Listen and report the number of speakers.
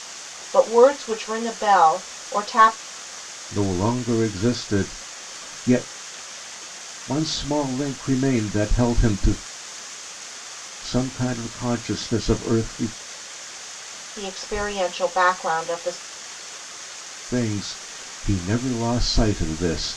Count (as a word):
two